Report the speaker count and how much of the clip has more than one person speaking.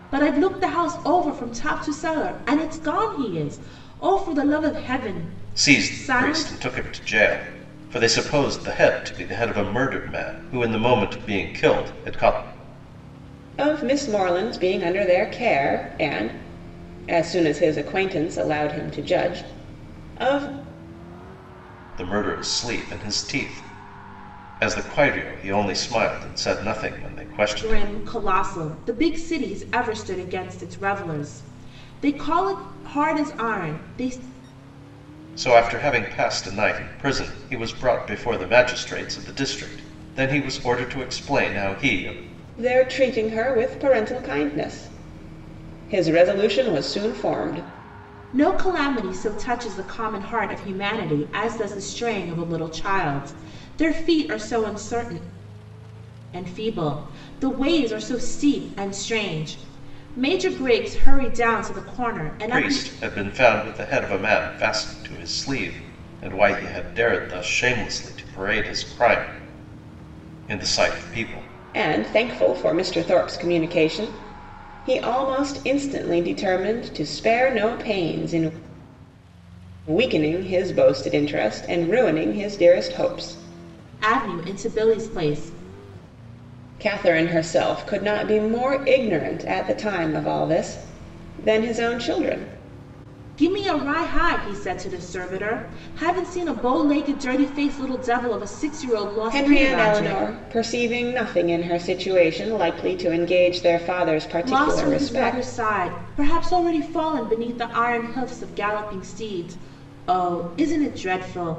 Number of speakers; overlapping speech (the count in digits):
3, about 4%